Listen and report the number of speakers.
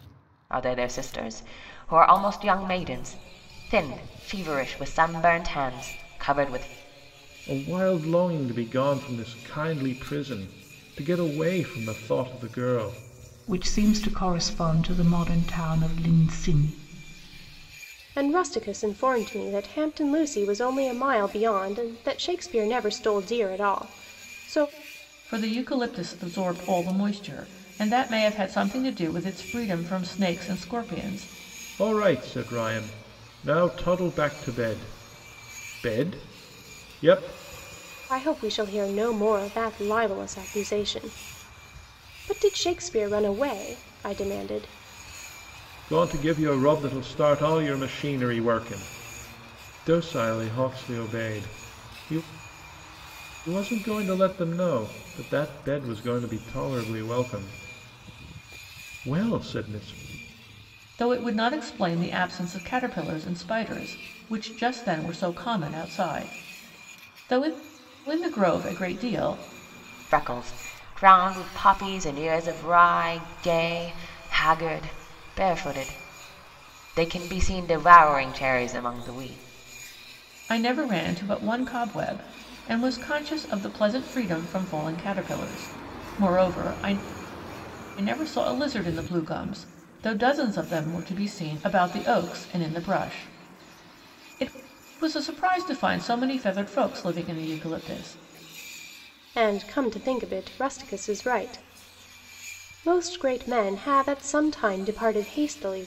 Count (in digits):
5